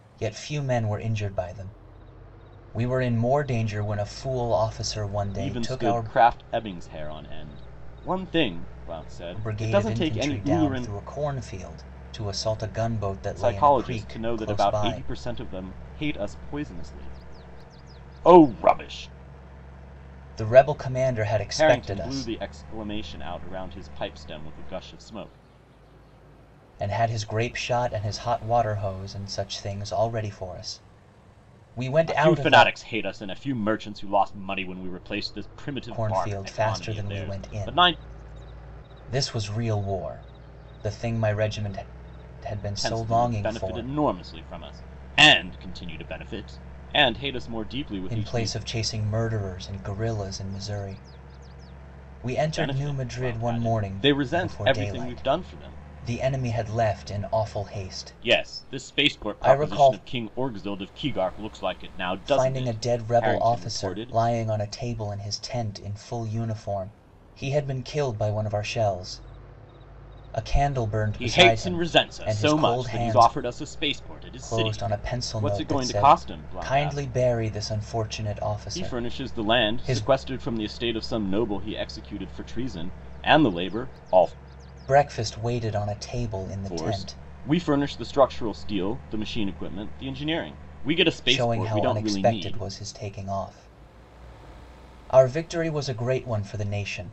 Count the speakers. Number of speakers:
two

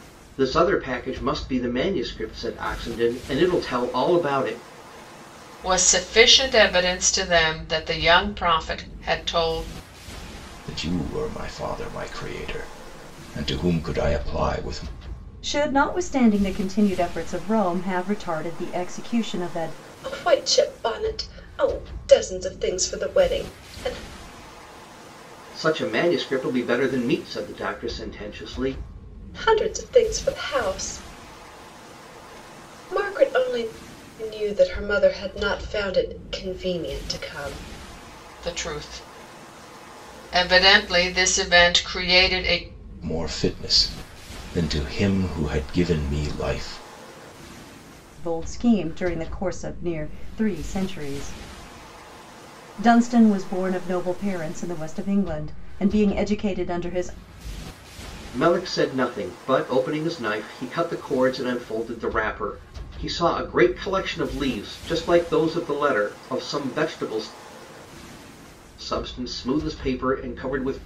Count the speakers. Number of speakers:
five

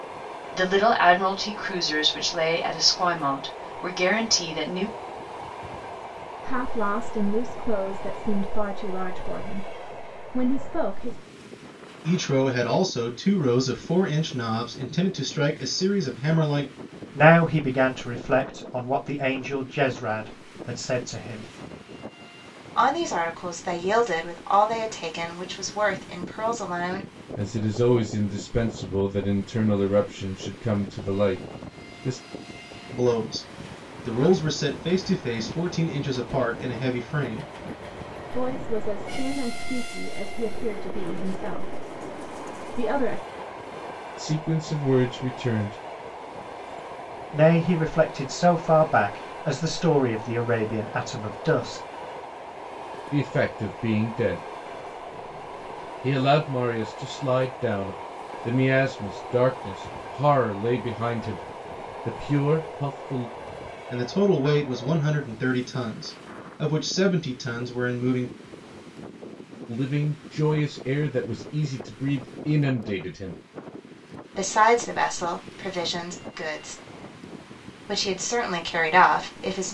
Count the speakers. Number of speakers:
six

